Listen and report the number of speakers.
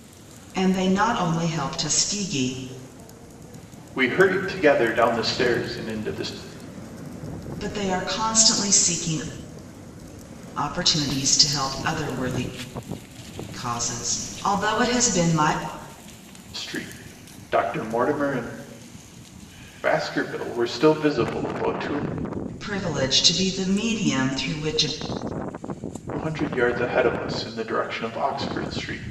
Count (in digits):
2